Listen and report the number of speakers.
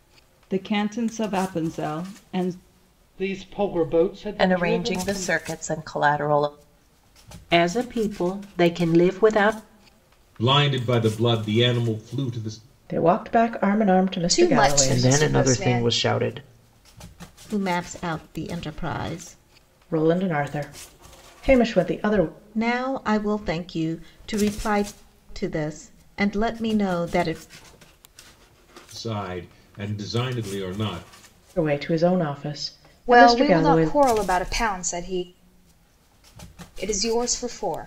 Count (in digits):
9